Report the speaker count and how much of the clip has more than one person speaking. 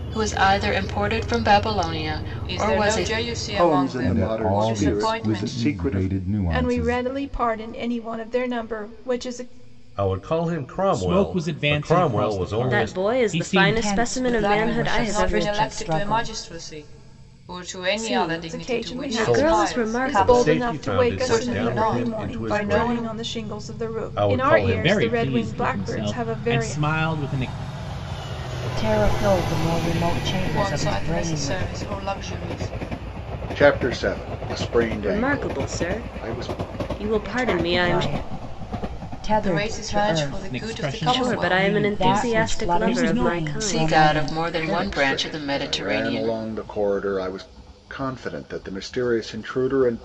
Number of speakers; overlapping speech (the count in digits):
9, about 58%